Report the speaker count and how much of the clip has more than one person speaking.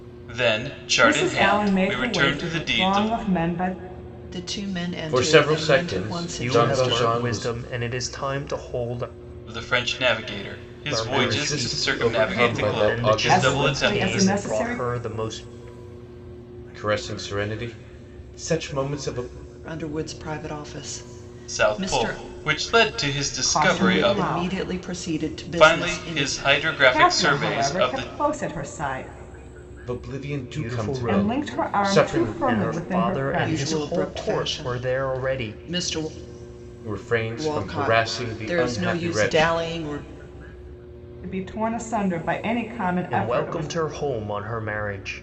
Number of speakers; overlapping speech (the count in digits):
5, about 46%